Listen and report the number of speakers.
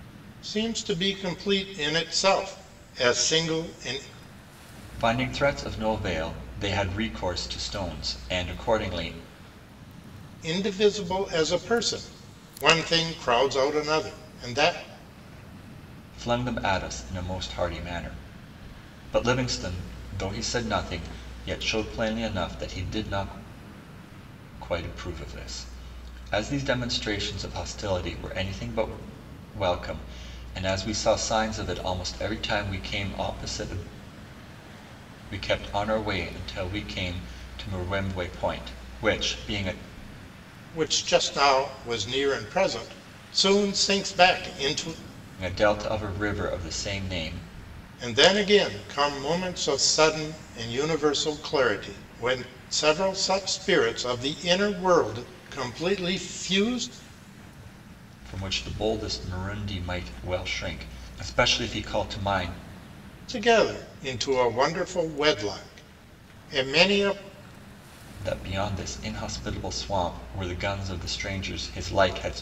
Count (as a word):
two